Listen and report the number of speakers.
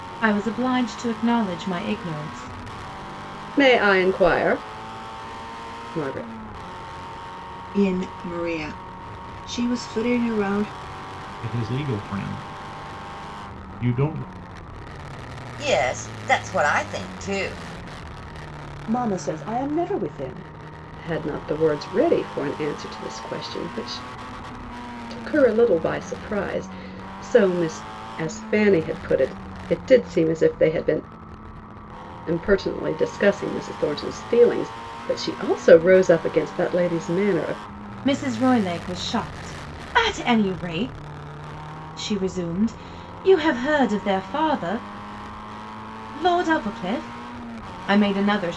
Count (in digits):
6